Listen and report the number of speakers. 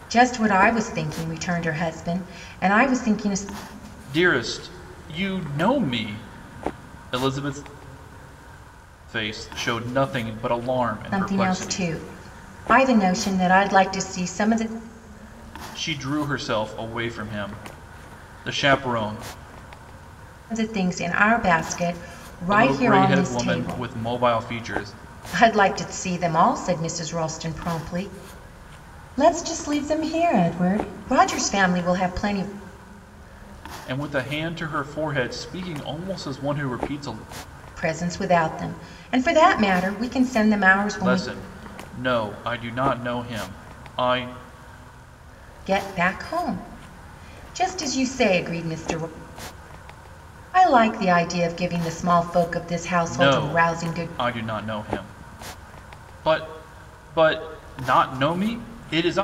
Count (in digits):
2